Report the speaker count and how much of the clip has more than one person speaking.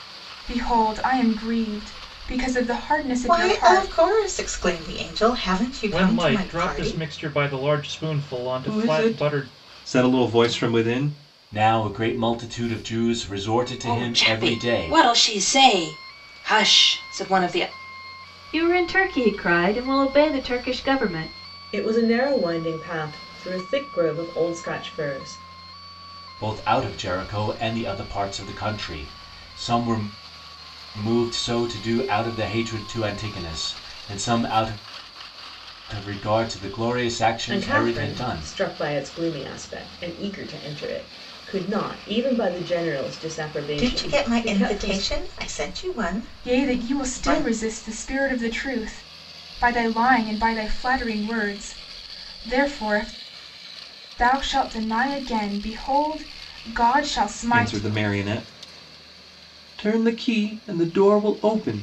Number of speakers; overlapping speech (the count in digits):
8, about 13%